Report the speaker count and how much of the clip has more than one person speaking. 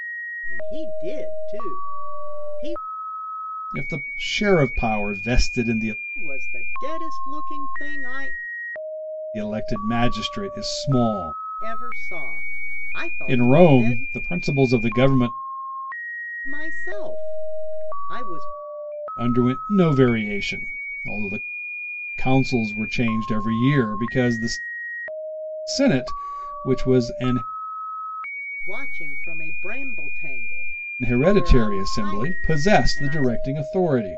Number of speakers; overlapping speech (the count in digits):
2, about 8%